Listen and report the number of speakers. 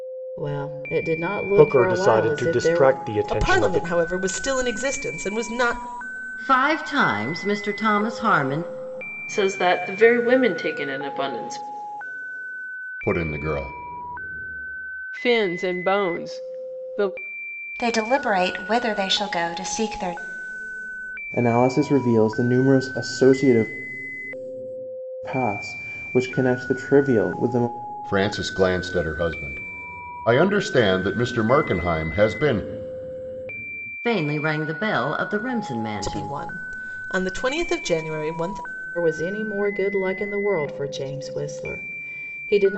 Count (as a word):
nine